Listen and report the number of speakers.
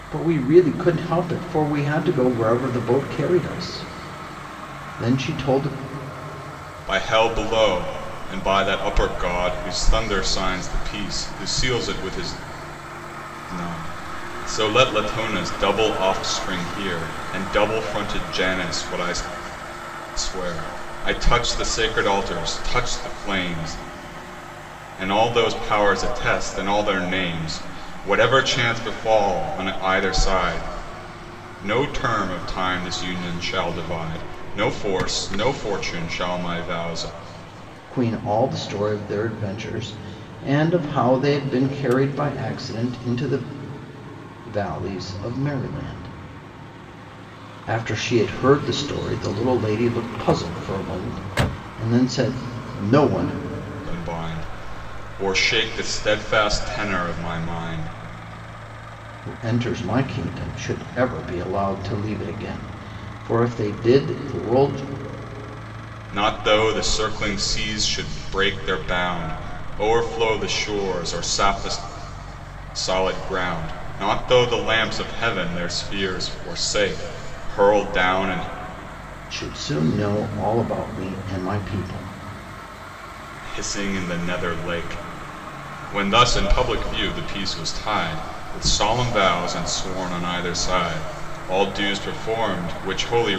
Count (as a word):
two